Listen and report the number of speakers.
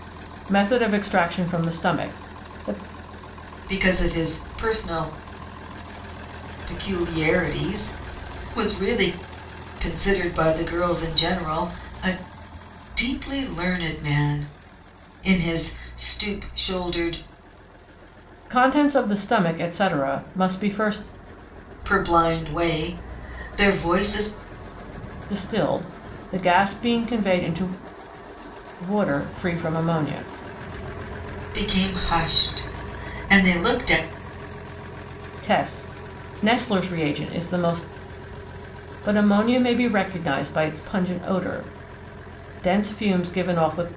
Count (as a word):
two